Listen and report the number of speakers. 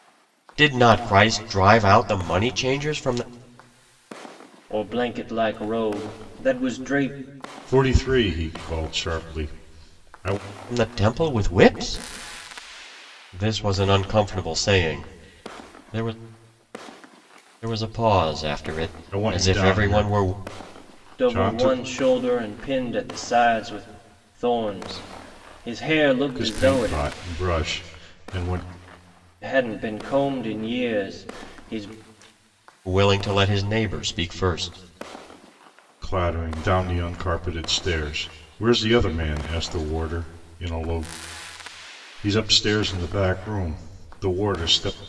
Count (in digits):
3